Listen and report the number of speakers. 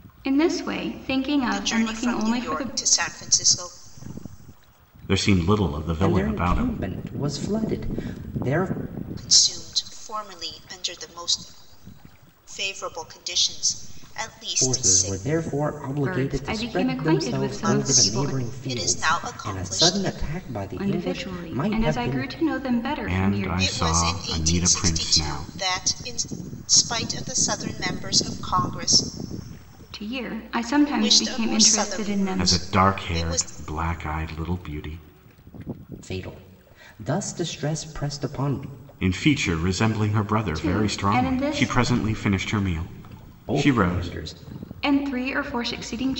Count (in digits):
4